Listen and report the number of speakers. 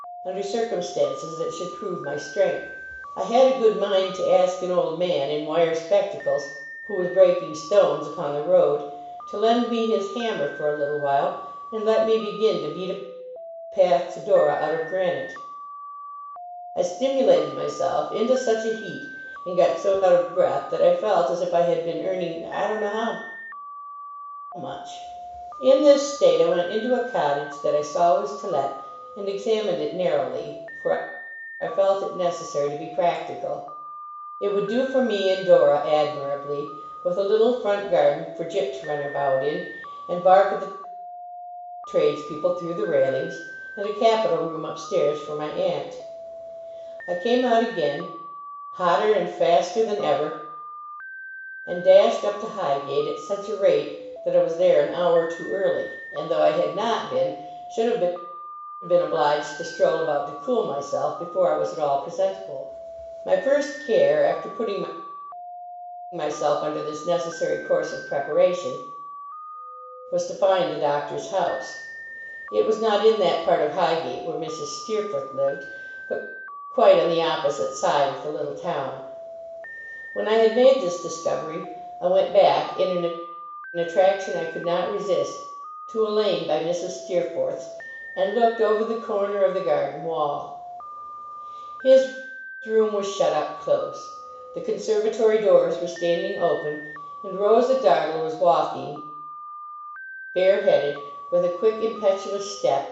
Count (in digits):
1